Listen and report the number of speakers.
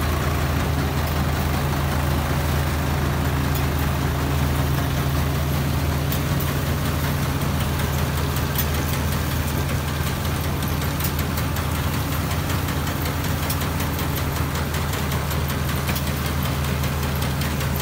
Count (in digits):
0